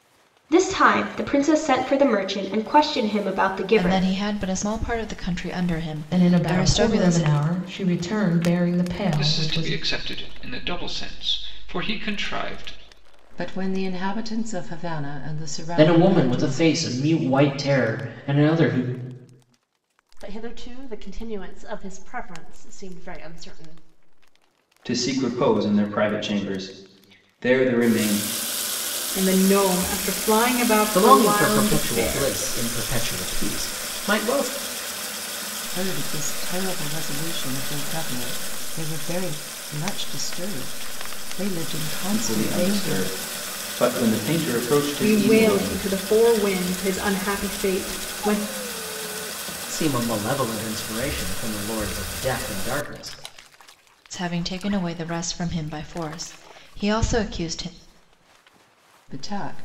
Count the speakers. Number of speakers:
10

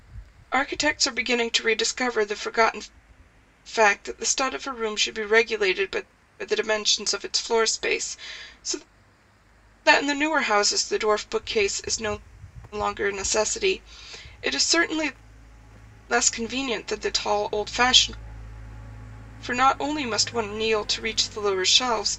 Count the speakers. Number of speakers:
1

